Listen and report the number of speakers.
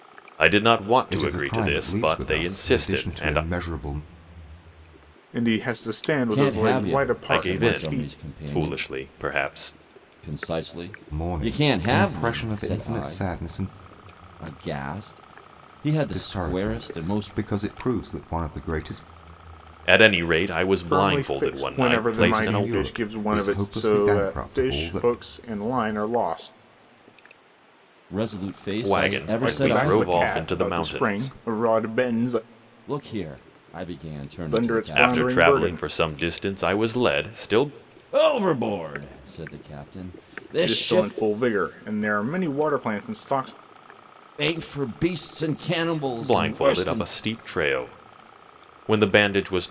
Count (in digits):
4